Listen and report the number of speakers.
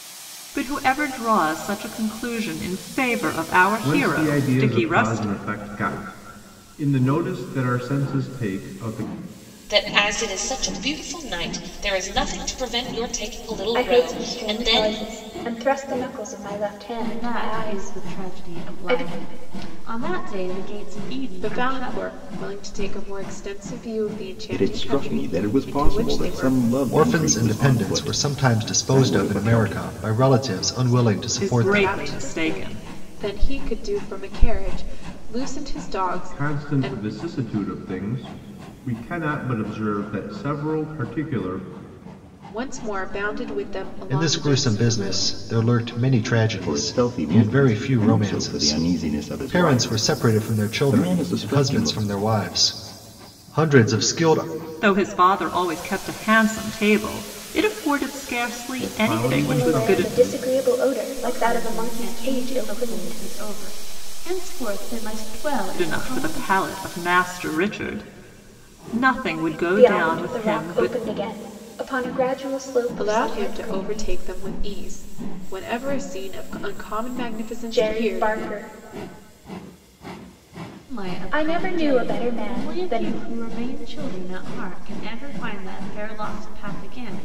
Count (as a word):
eight